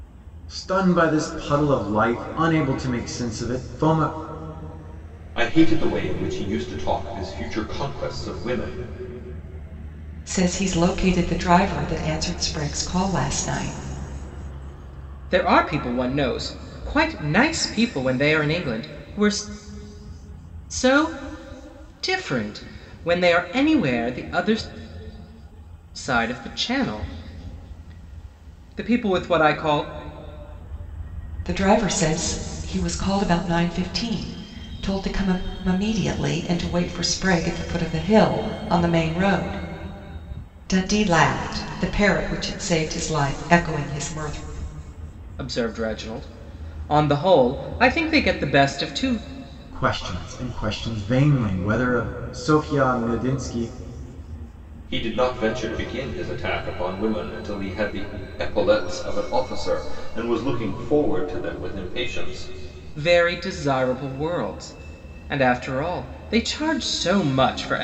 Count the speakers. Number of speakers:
4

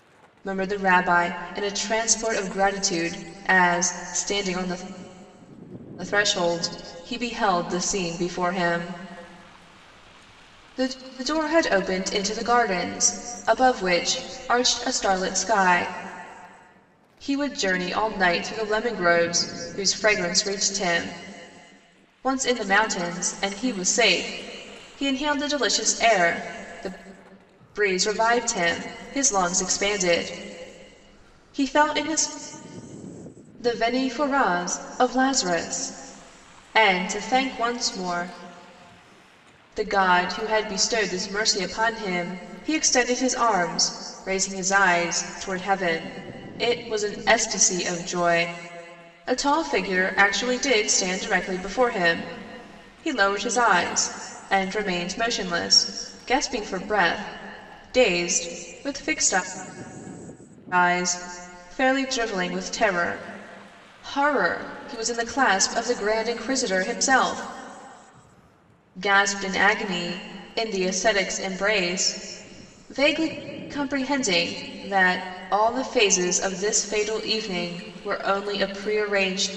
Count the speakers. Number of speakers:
1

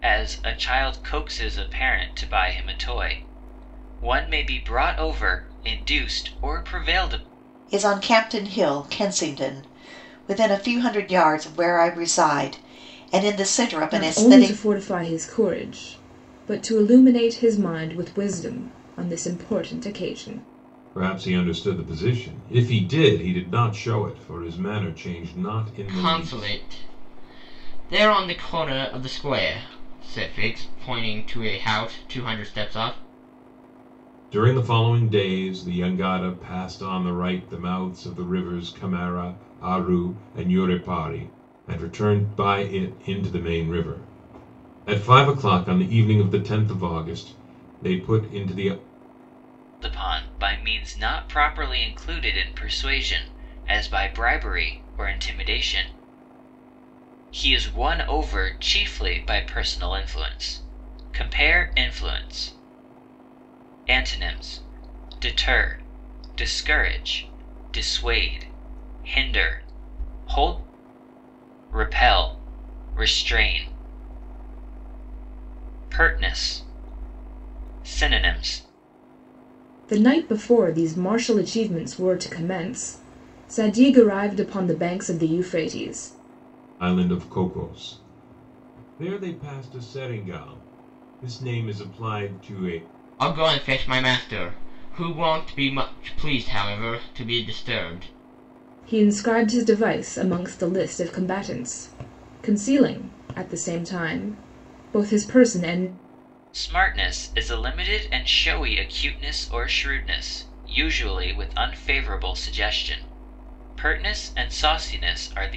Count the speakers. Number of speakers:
5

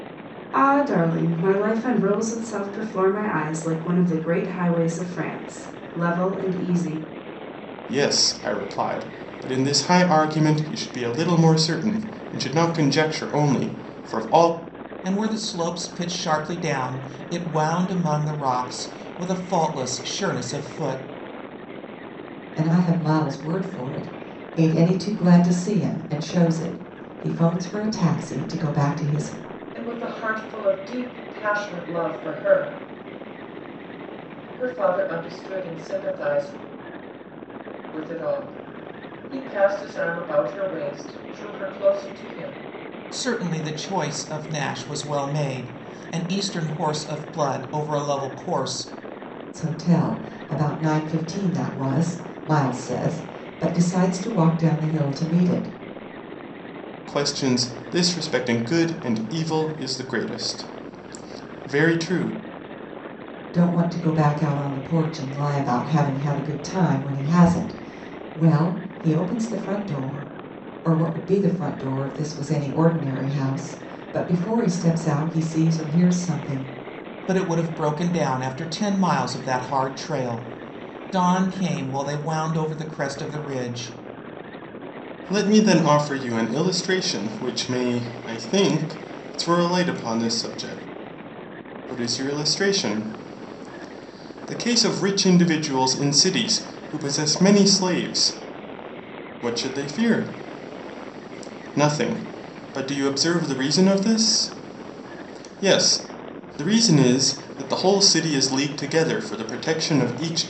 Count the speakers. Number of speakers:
5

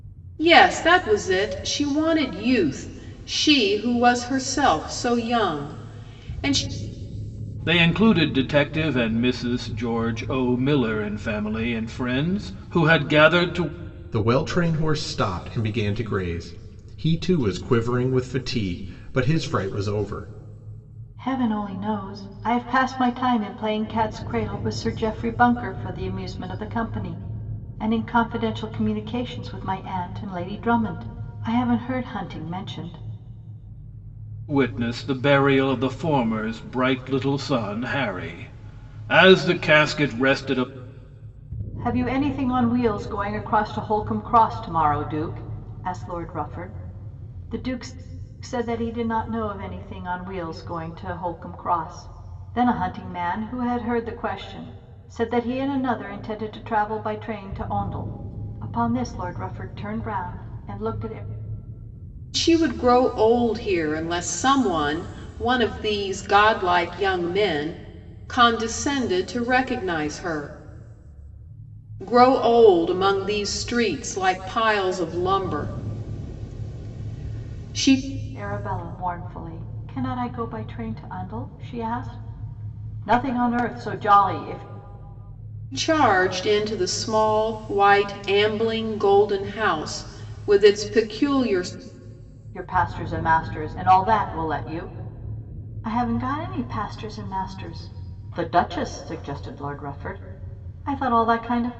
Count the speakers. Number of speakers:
4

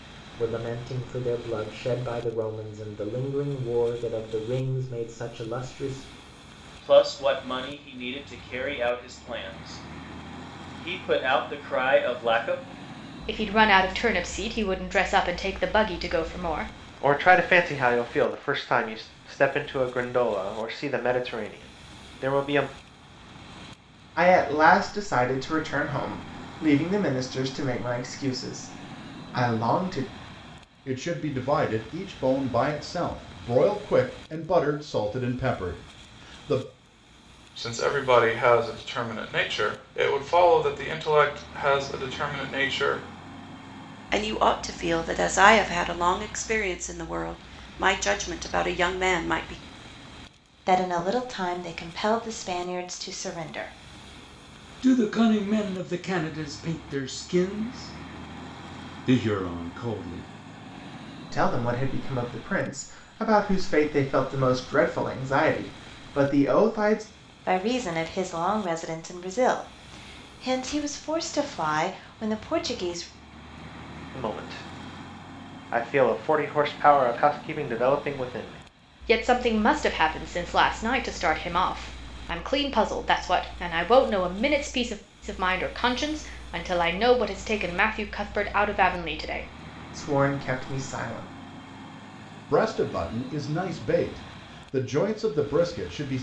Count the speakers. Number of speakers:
10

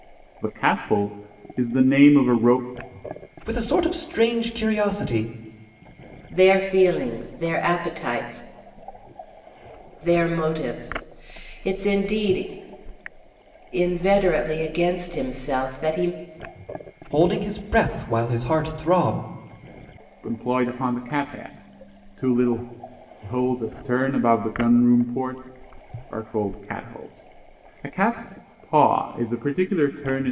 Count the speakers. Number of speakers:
3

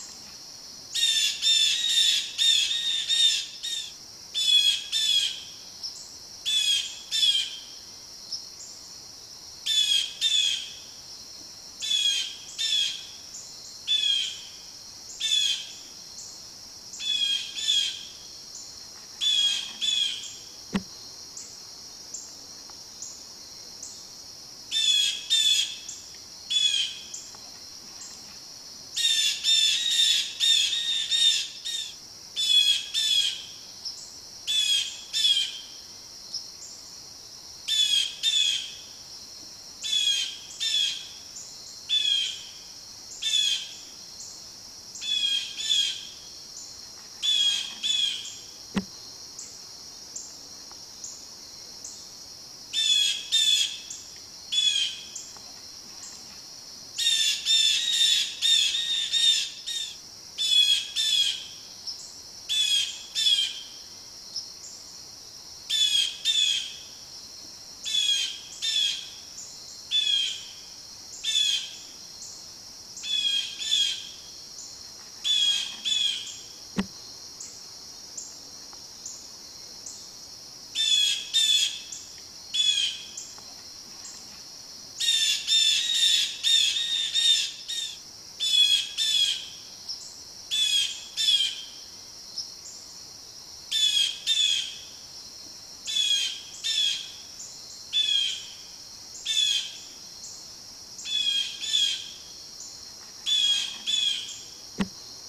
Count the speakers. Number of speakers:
0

